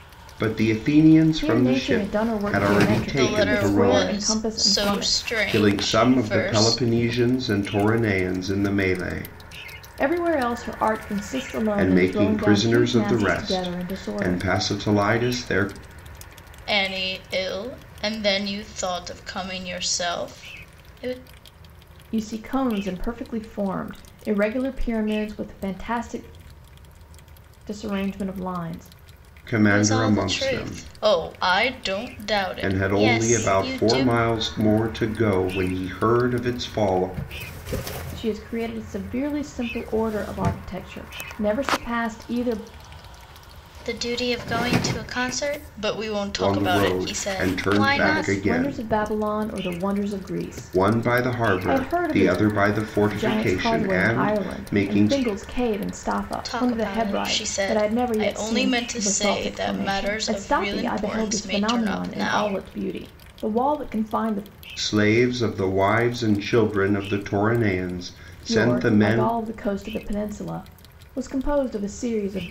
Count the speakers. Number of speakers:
3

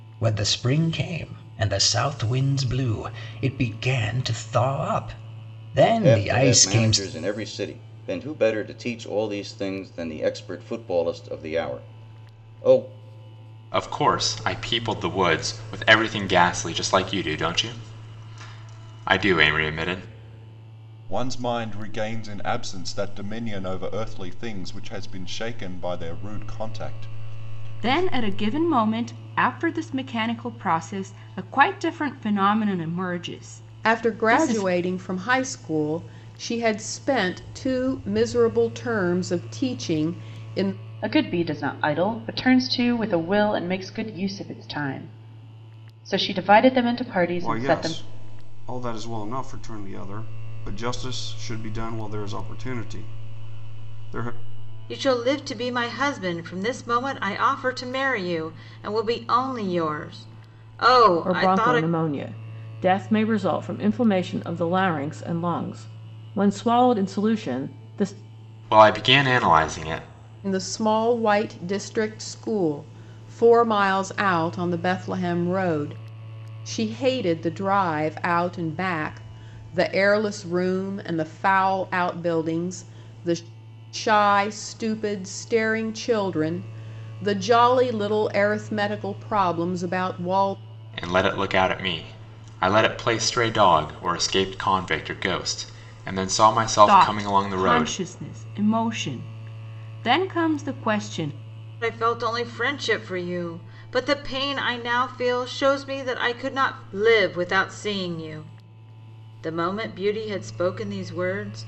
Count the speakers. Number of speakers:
10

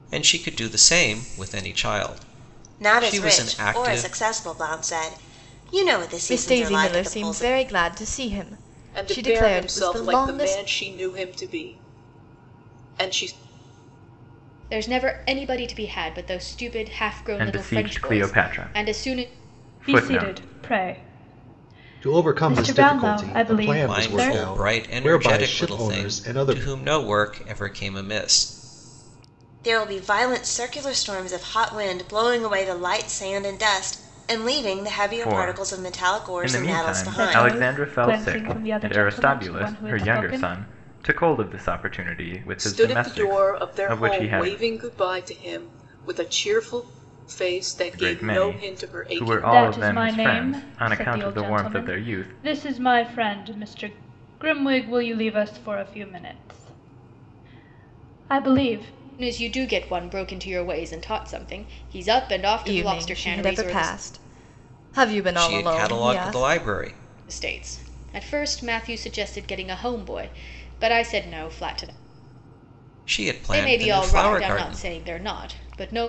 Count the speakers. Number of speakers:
8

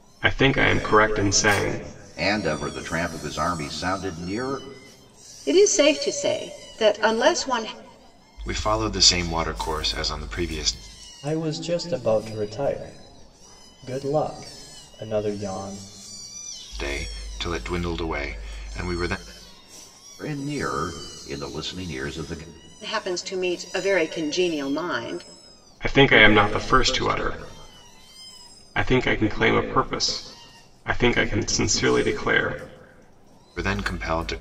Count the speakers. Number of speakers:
5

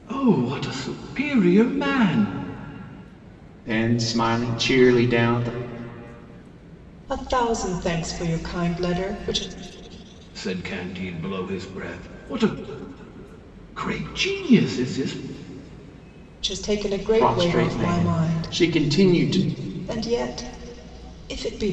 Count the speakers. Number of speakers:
3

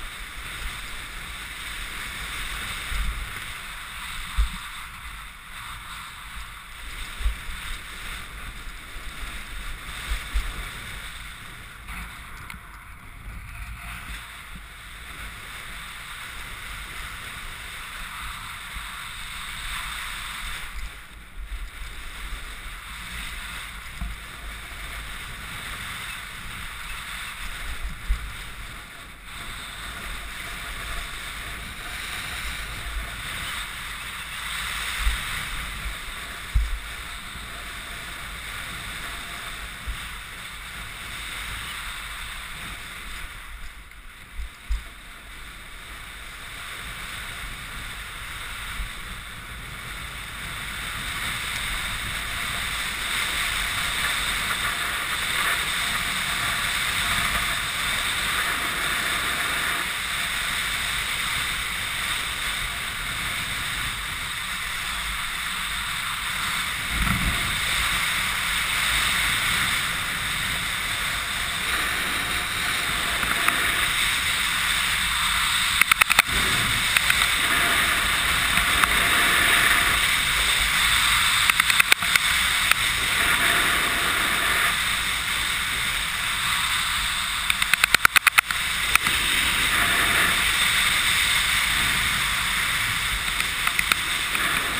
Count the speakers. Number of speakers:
0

